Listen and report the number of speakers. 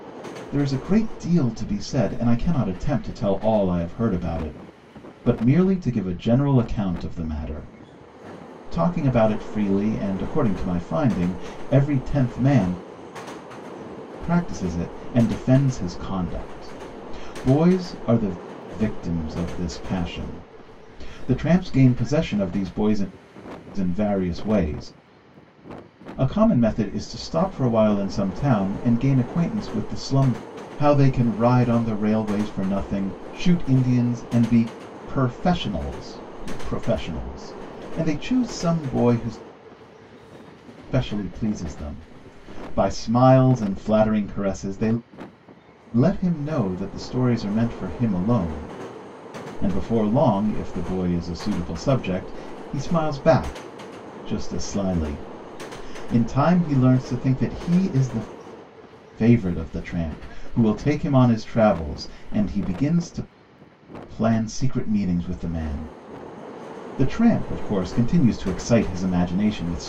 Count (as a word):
one